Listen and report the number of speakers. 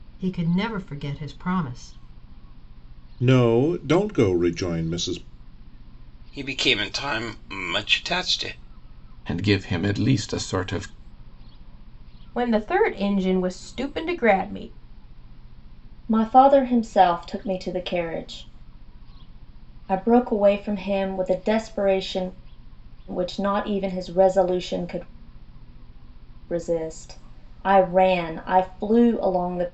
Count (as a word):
six